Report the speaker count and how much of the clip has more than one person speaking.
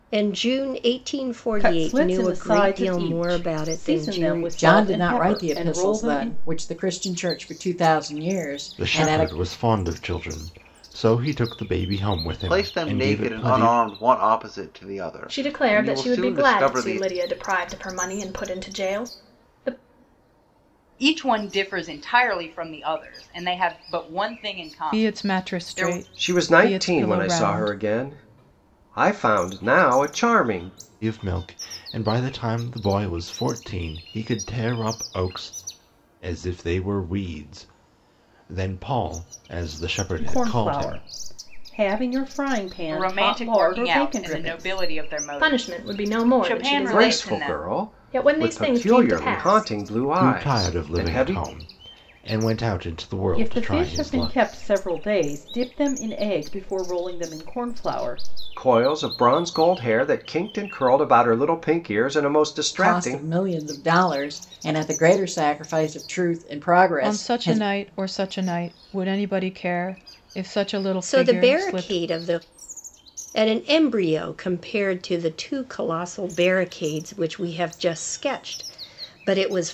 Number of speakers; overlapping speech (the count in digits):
9, about 30%